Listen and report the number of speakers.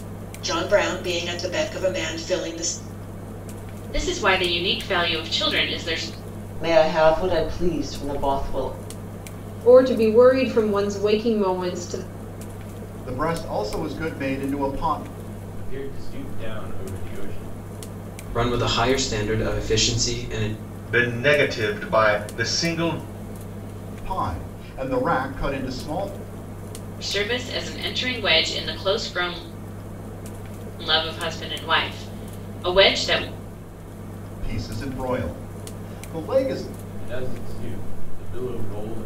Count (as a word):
eight